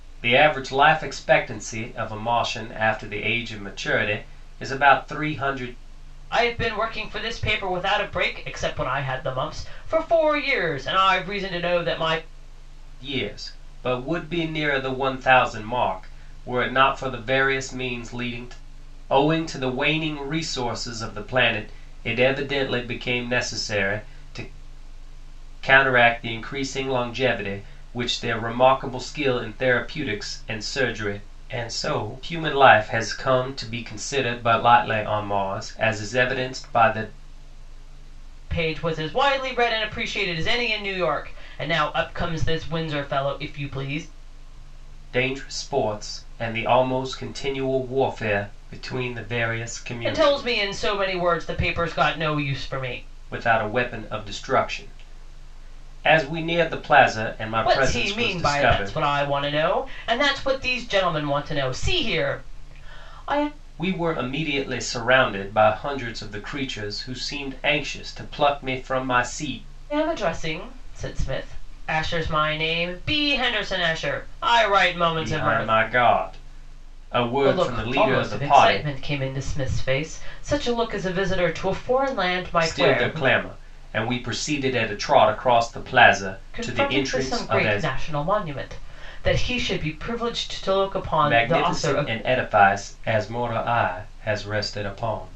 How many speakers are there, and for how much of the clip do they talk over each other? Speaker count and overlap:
two, about 8%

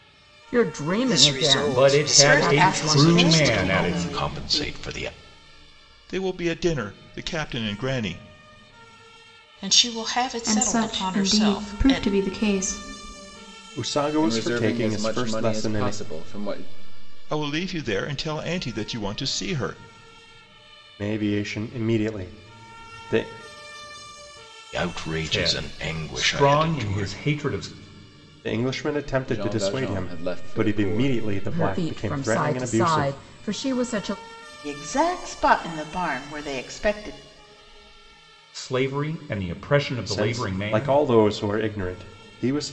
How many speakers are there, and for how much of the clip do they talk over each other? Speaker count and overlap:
ten, about 32%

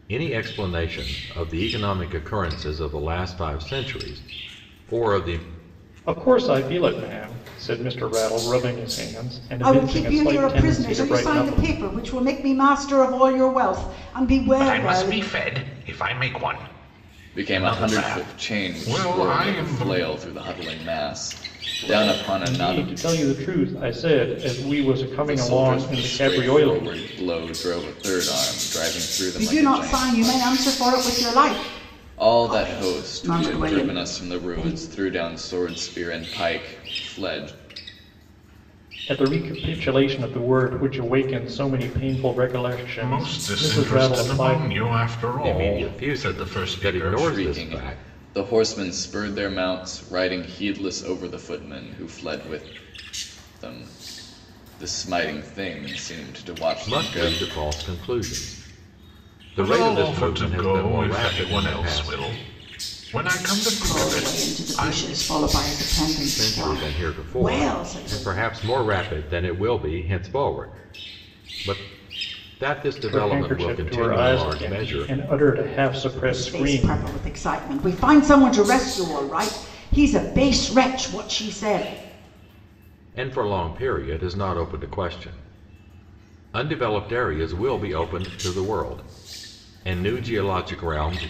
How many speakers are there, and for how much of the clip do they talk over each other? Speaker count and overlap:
five, about 29%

